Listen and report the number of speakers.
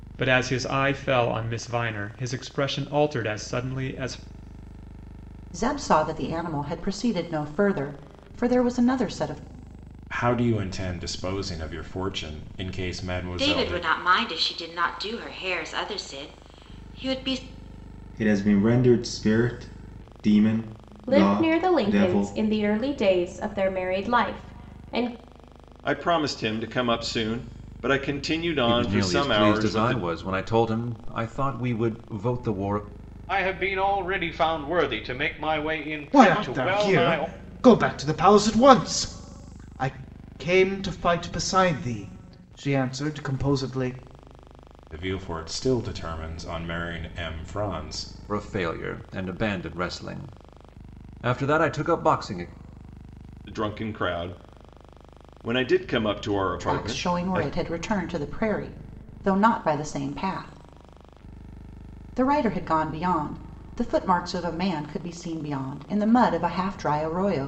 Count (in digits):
10